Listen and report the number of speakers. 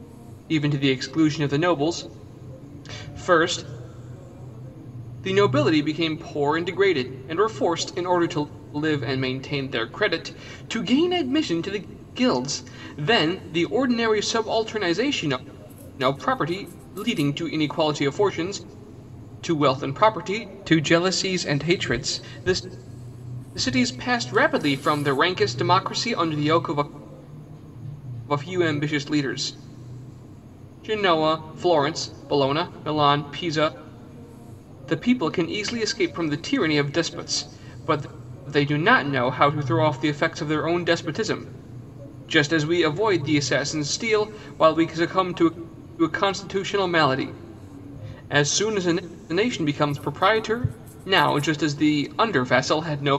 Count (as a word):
one